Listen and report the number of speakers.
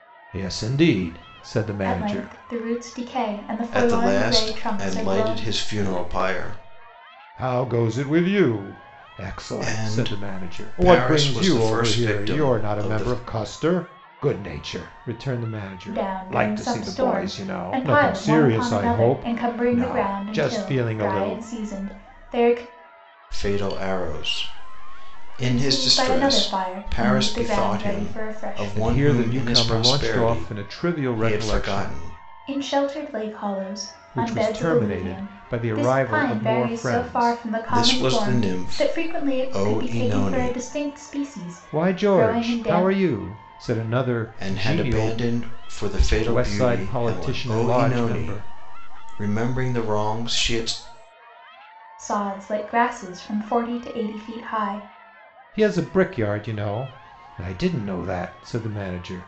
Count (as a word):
three